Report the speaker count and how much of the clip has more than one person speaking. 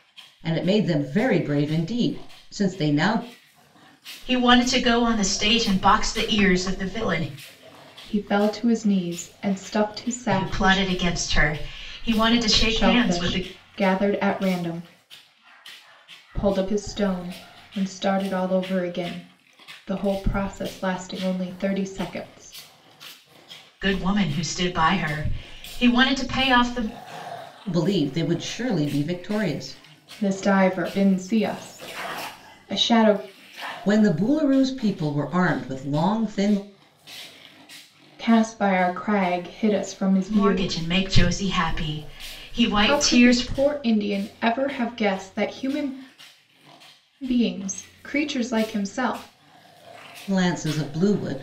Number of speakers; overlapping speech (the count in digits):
3, about 5%